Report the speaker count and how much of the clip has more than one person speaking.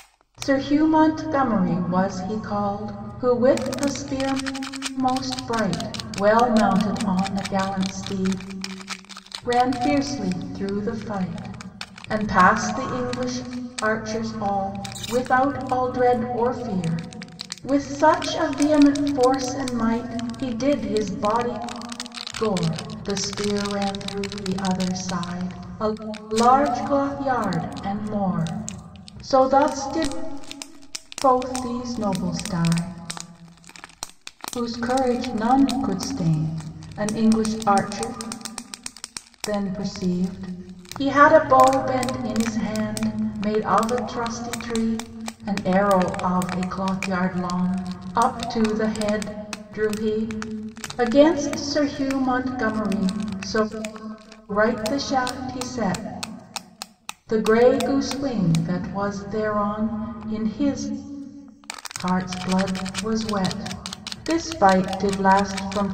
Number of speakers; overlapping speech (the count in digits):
1, no overlap